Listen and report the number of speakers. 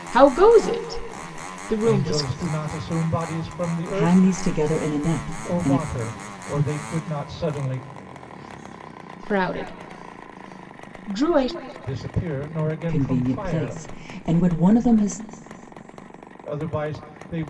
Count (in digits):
3